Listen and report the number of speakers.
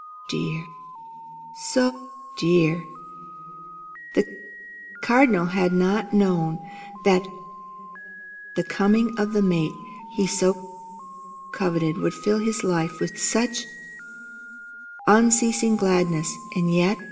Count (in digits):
1